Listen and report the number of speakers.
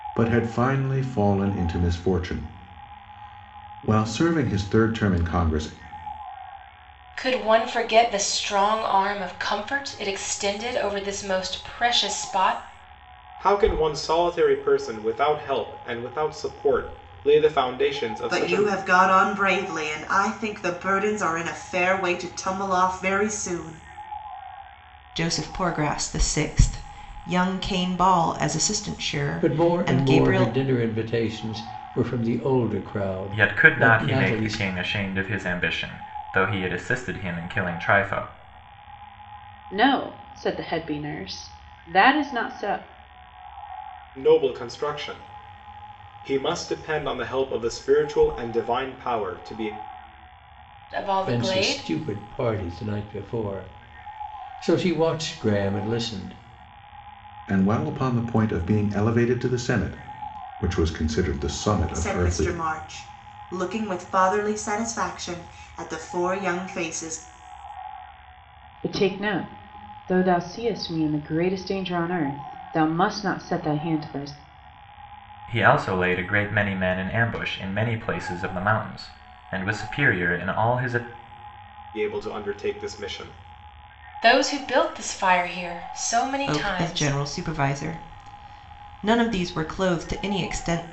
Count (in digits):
8